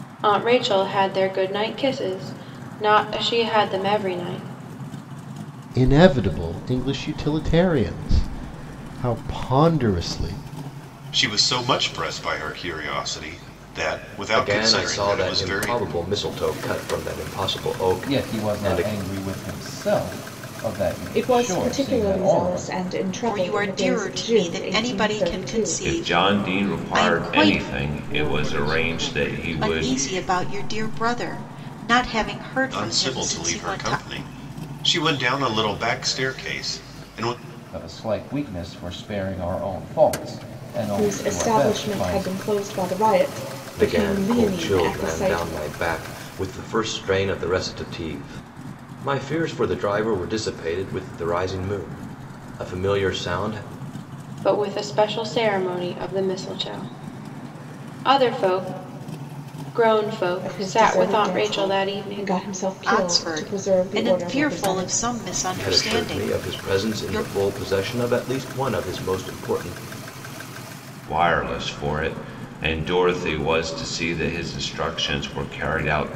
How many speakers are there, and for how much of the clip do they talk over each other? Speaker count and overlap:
9, about 28%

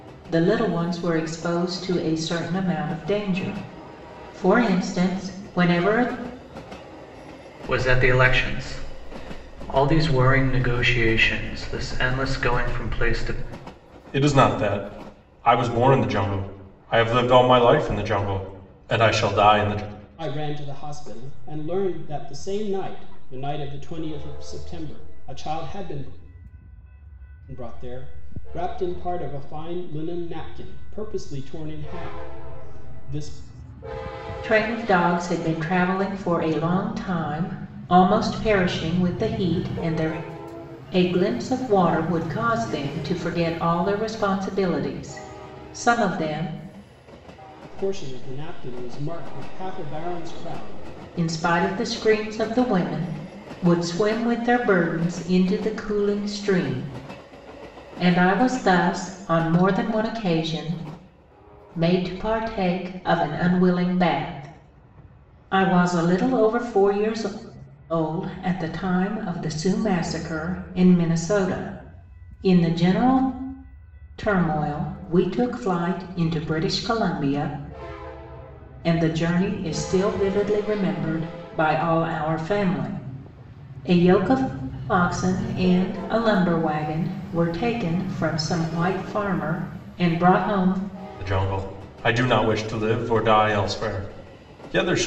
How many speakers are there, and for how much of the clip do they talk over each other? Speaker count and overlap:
4, no overlap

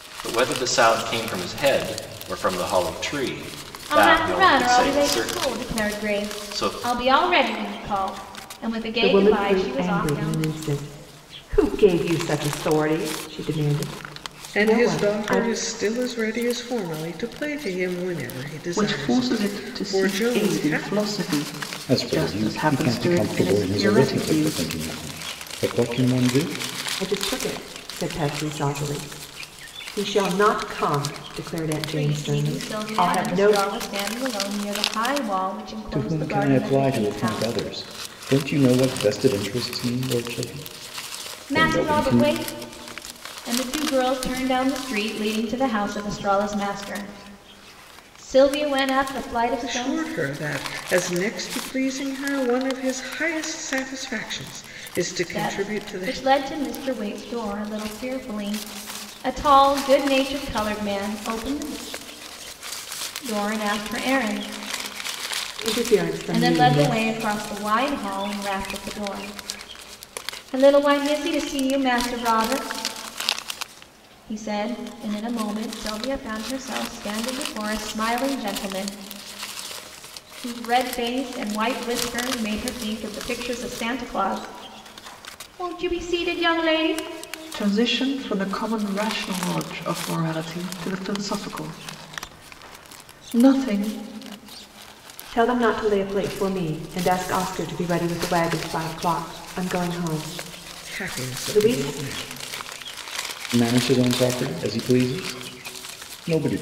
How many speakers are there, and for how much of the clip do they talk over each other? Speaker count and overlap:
6, about 17%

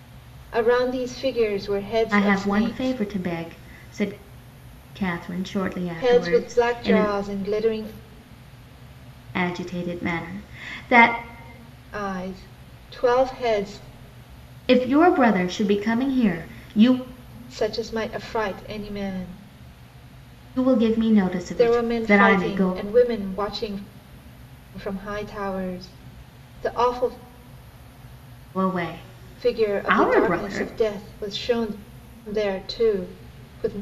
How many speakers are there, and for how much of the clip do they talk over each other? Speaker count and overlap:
2, about 14%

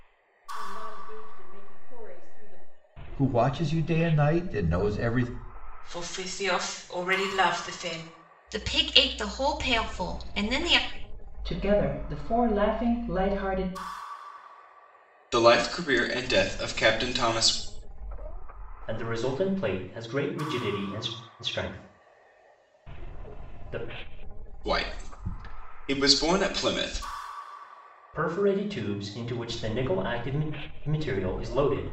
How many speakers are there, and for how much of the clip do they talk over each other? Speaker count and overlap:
7, no overlap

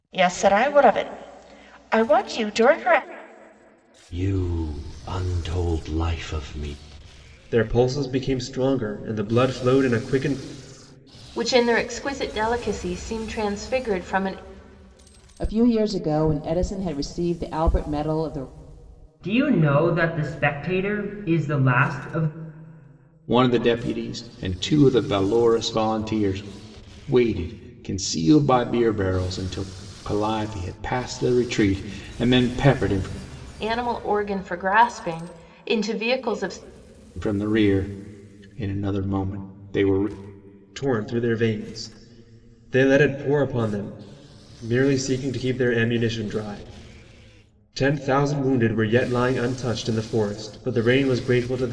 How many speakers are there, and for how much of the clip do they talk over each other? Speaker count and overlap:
7, no overlap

